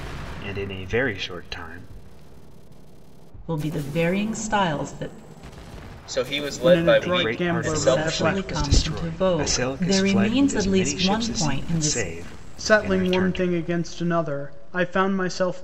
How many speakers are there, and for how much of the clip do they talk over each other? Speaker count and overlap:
four, about 41%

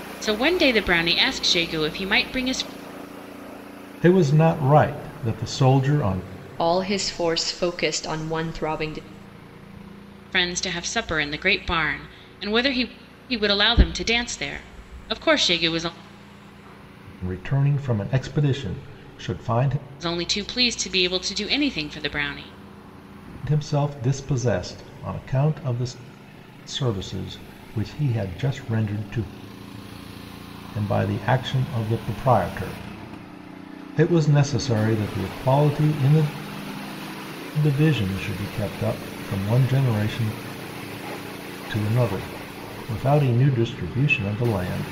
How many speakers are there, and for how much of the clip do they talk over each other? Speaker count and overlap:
three, no overlap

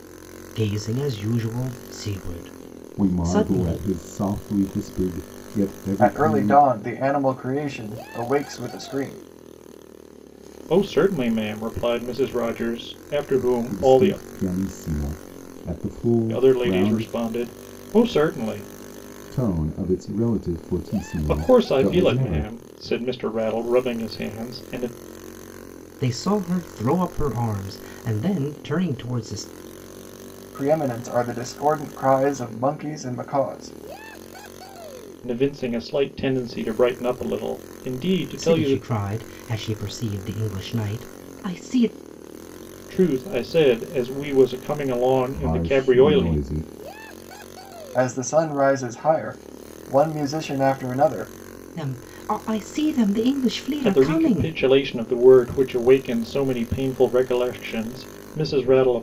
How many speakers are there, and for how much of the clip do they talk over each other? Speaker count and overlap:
four, about 11%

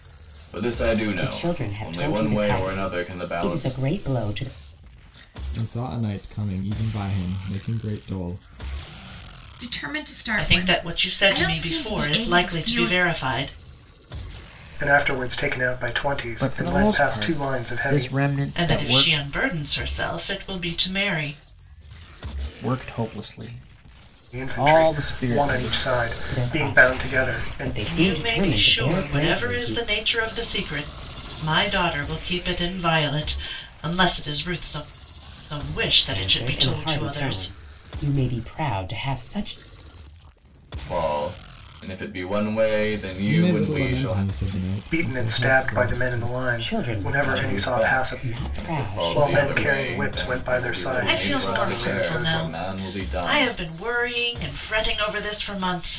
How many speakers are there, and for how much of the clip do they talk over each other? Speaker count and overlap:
seven, about 43%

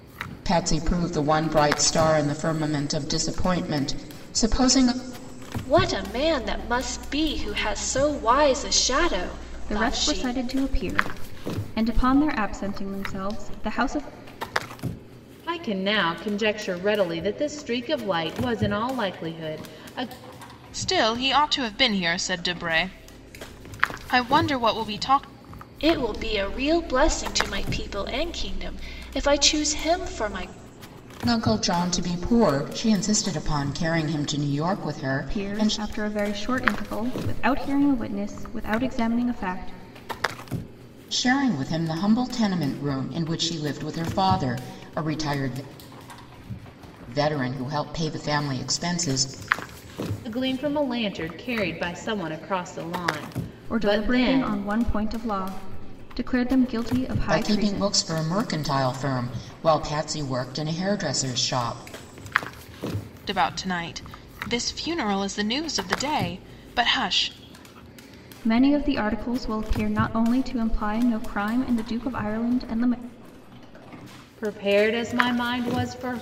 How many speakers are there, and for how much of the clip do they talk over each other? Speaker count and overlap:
five, about 4%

